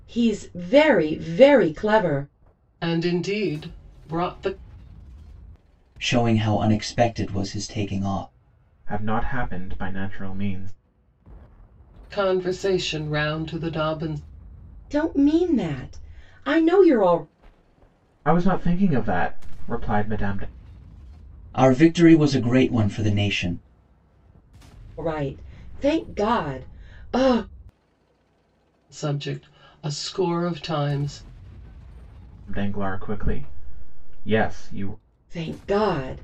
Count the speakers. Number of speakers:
4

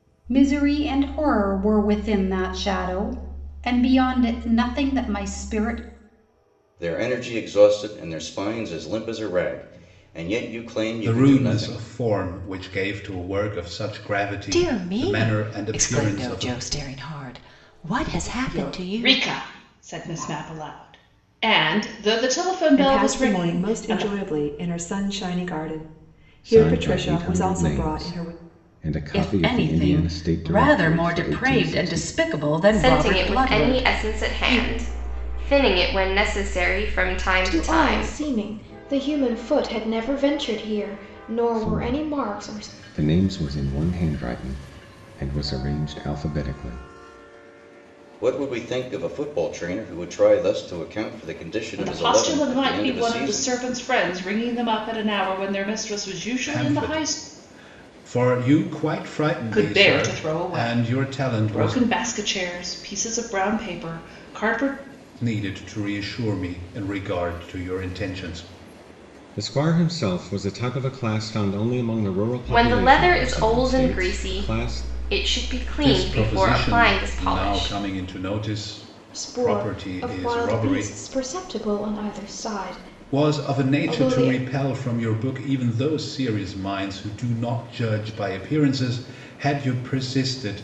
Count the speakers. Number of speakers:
10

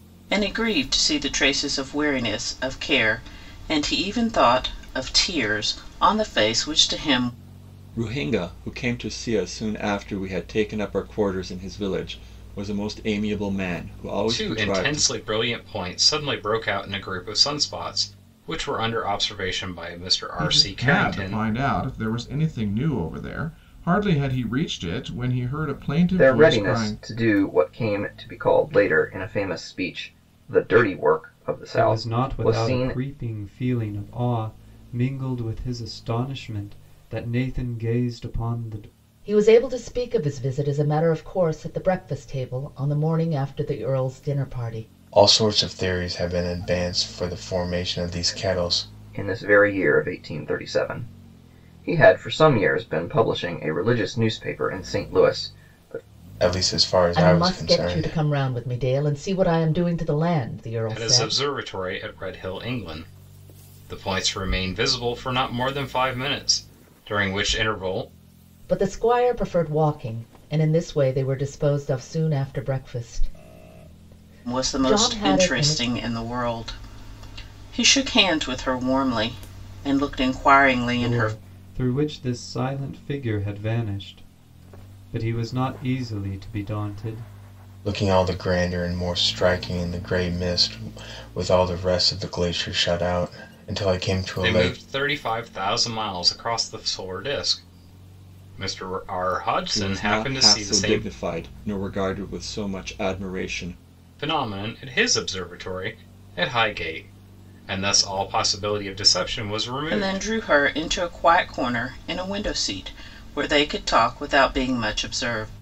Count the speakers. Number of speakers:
8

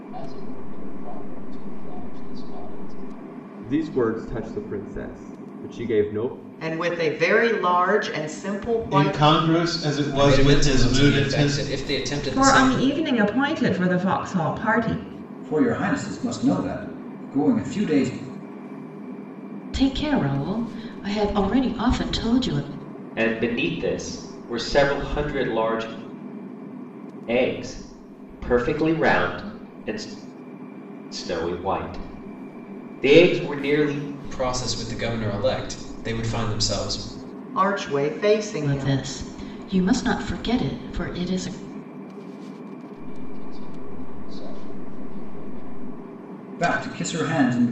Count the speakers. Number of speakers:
9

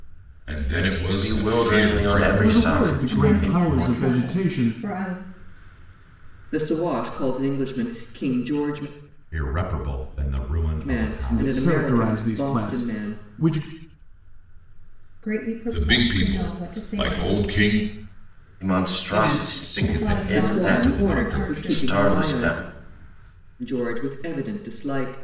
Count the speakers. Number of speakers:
6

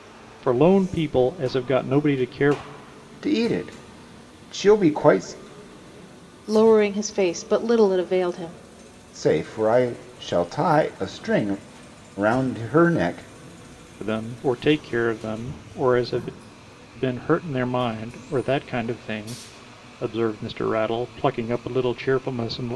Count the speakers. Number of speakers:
3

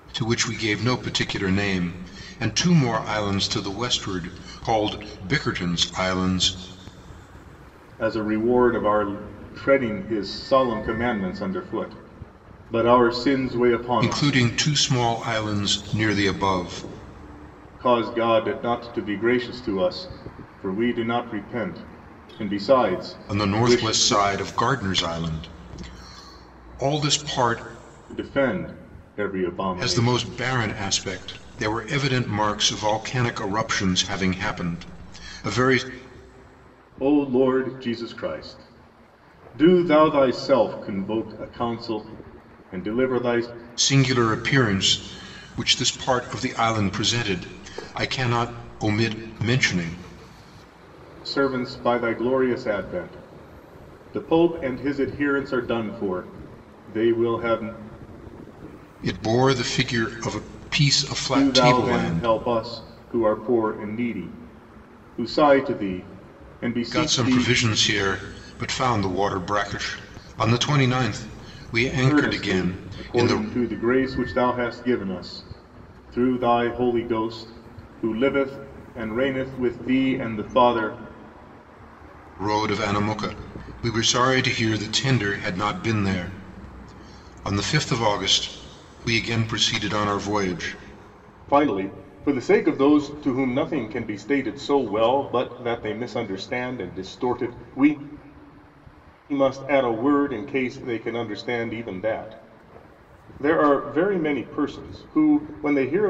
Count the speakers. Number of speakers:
2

